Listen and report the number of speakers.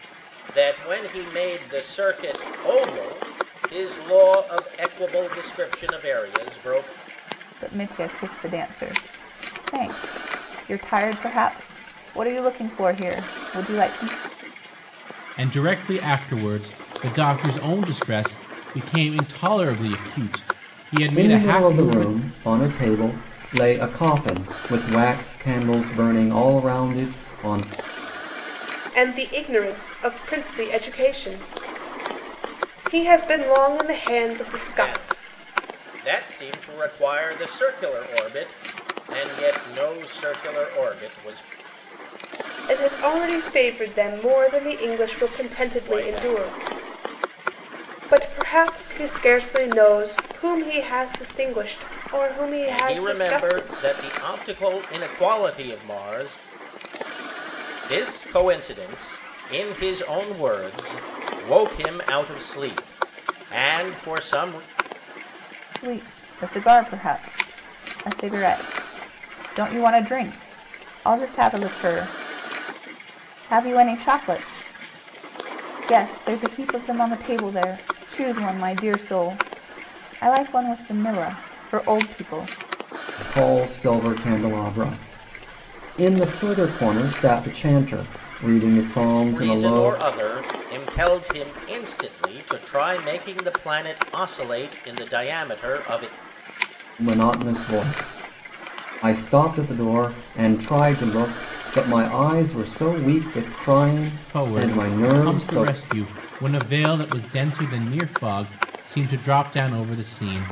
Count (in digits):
5